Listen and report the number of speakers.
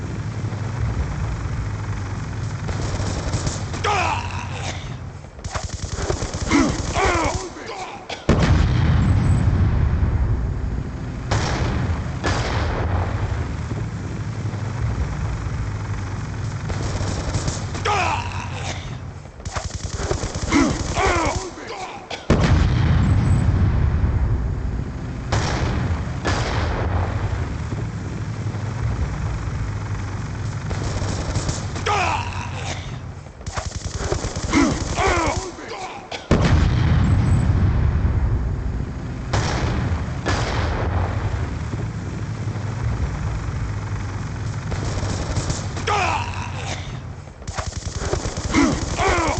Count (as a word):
zero